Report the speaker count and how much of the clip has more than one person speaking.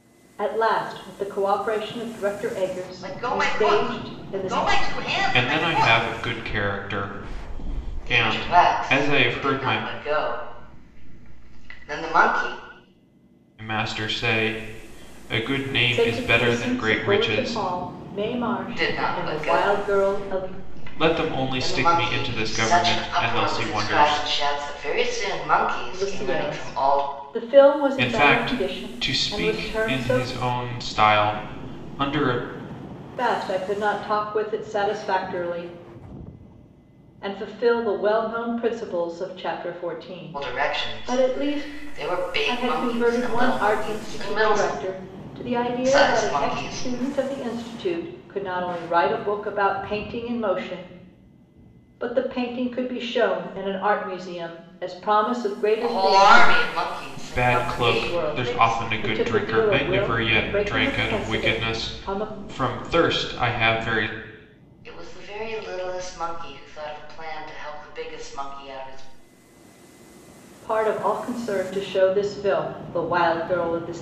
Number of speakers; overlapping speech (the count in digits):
3, about 34%